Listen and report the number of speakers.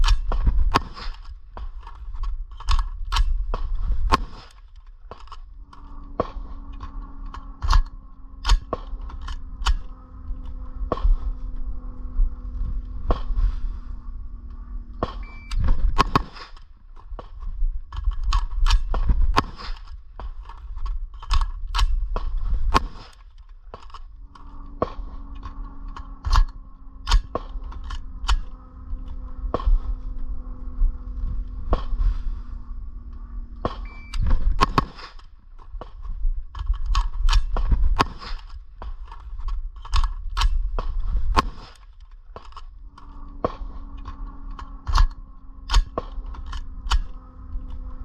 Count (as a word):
zero